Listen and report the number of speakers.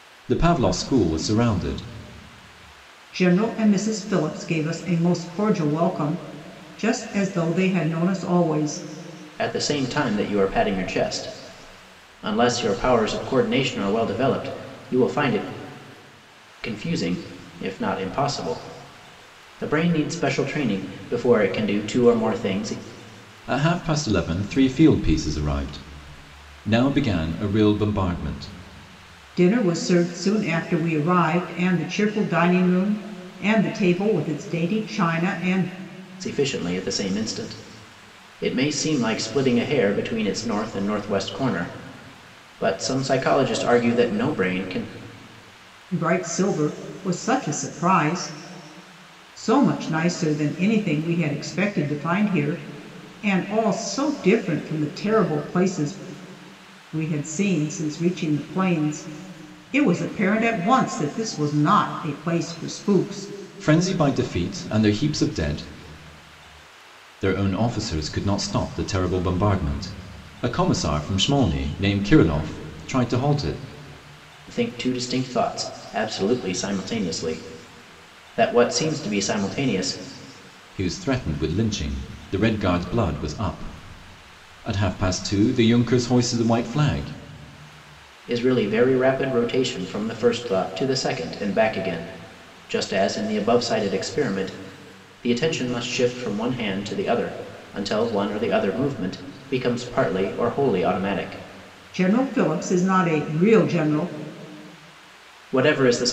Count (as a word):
three